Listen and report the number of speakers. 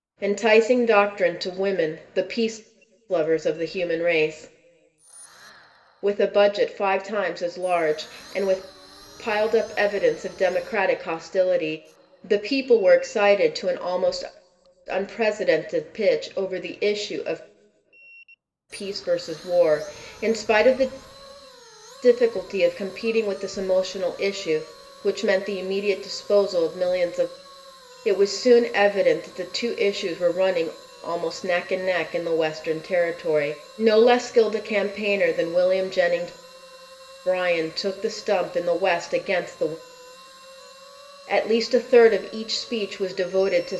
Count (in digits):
1